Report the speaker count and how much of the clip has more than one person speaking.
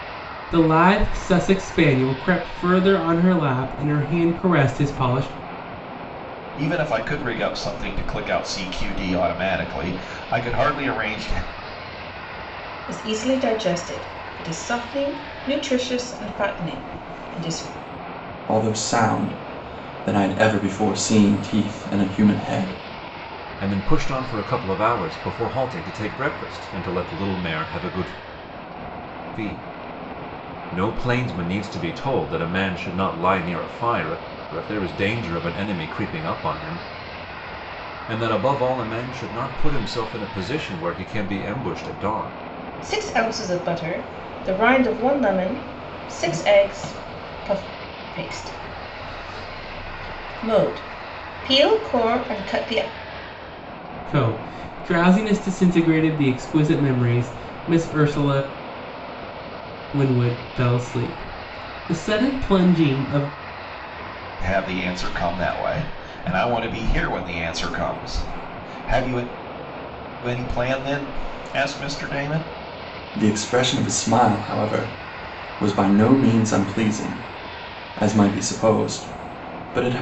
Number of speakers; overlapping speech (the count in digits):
5, no overlap